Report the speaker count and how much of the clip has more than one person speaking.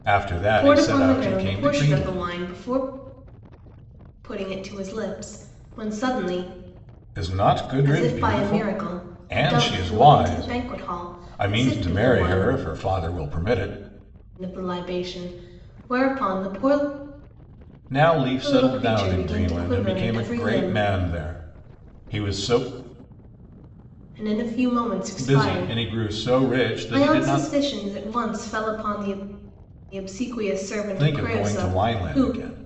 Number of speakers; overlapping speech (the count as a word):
two, about 34%